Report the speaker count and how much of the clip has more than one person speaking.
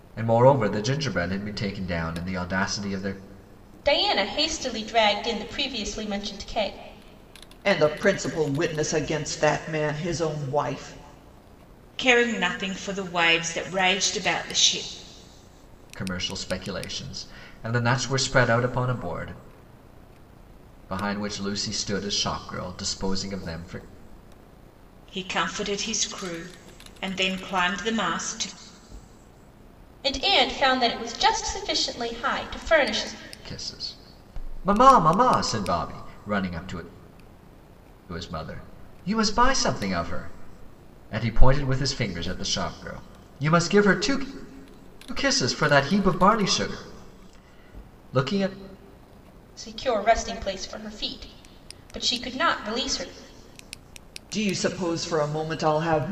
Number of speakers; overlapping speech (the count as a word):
four, no overlap